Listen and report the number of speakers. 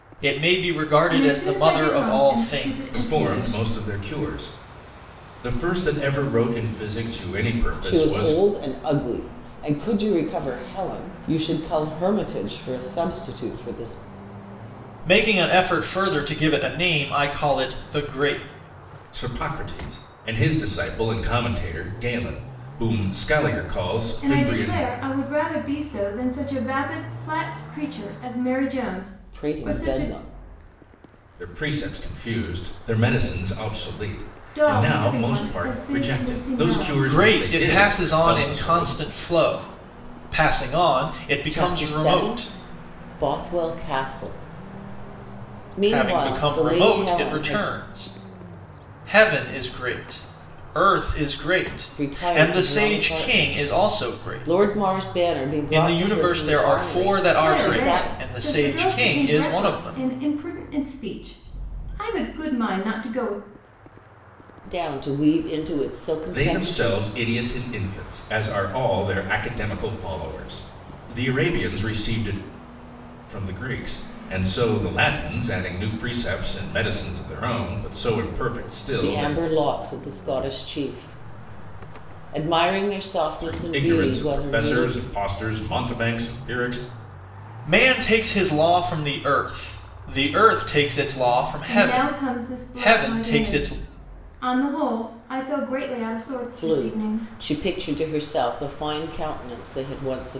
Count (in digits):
4